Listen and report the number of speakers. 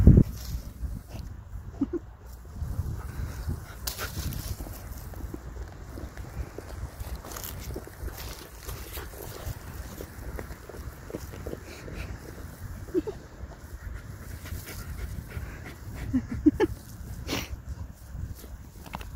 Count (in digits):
0